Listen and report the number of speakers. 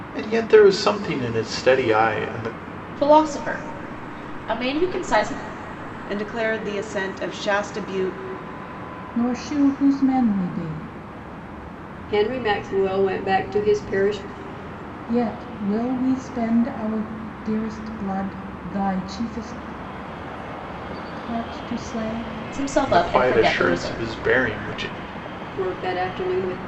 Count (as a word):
five